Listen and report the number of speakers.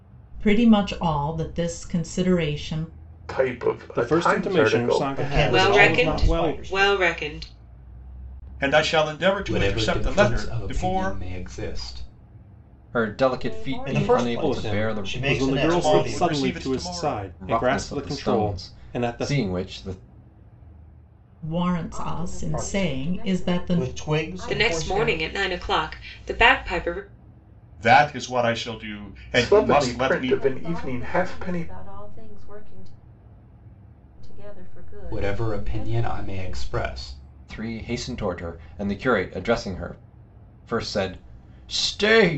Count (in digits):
9